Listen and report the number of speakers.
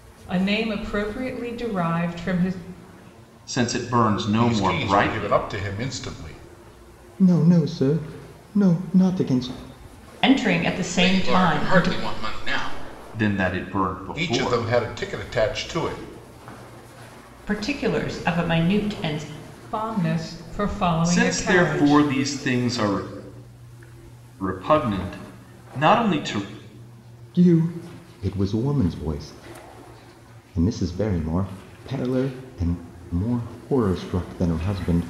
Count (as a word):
six